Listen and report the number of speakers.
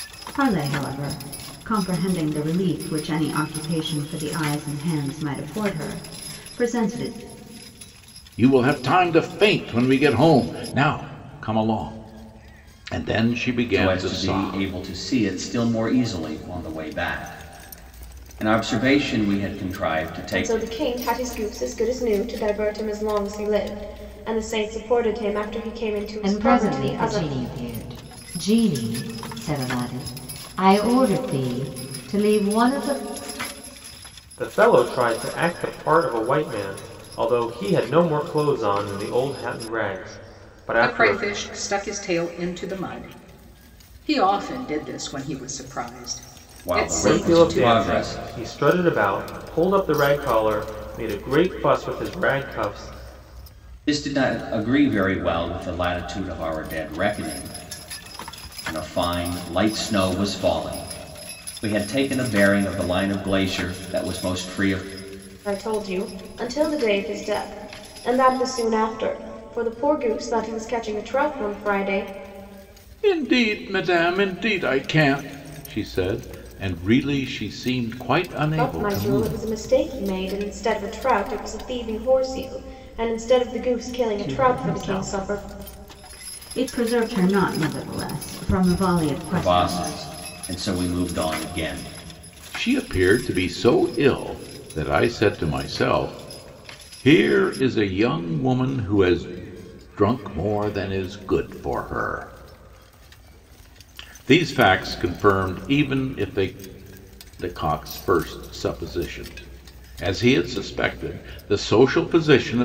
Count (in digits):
7